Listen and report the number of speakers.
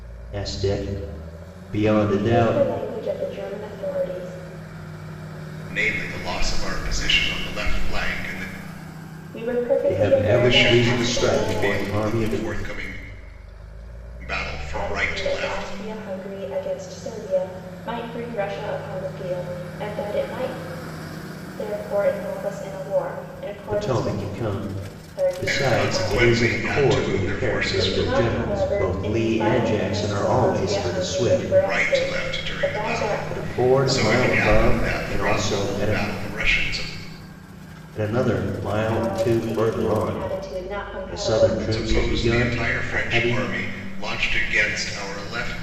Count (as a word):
three